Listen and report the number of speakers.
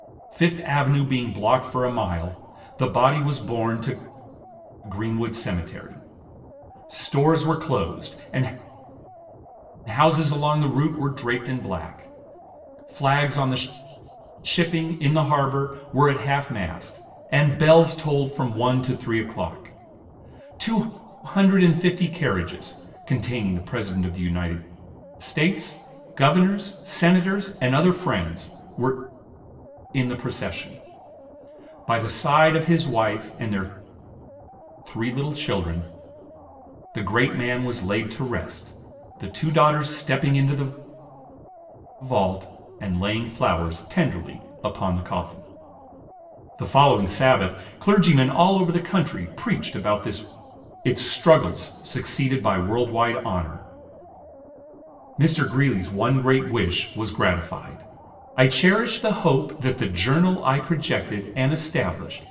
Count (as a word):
one